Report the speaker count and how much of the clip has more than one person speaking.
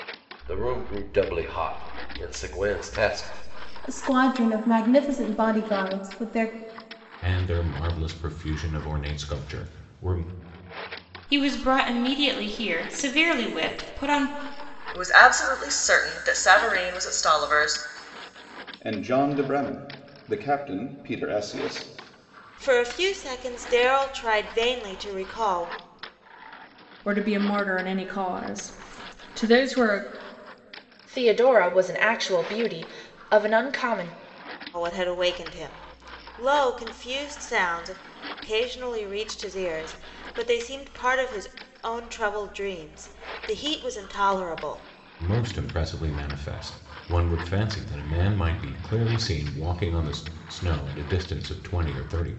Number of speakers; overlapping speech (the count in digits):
9, no overlap